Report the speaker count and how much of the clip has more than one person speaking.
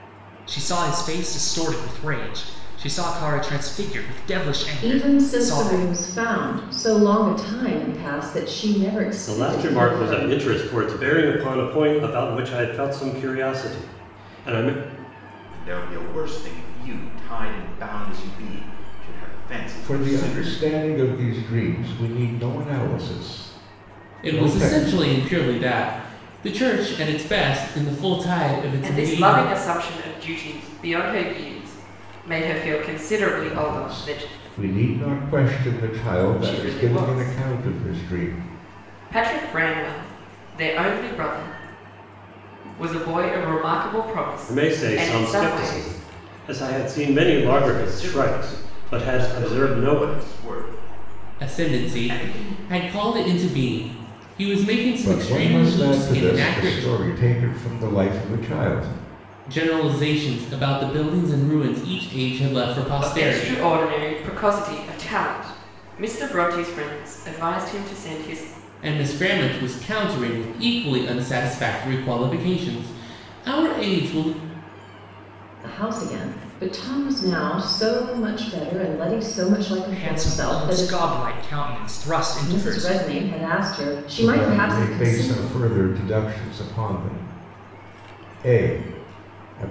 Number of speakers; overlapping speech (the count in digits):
7, about 21%